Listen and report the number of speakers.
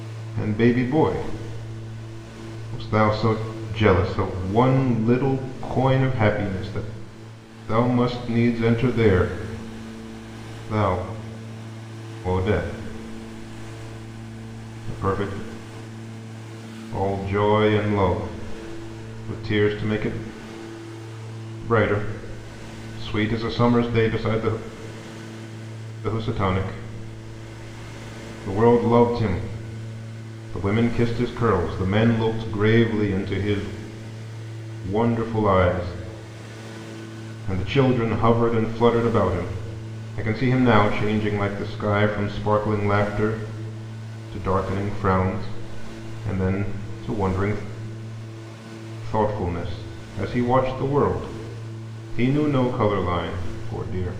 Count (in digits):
1